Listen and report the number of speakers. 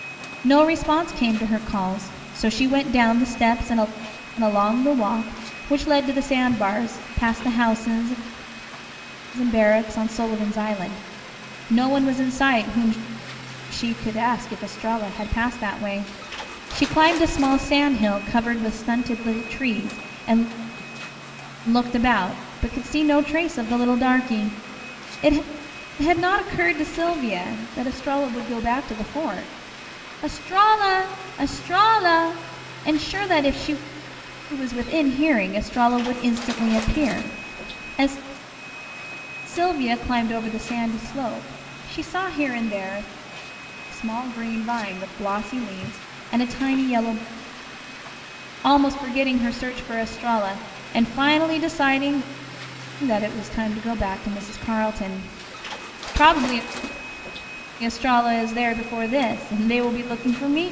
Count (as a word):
one